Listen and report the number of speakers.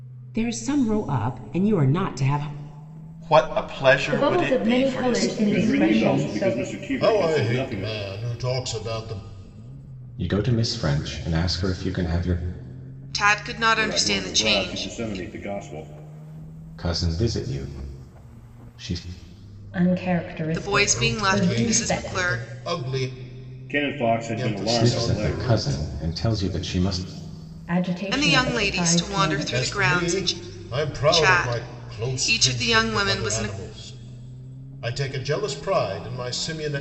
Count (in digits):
8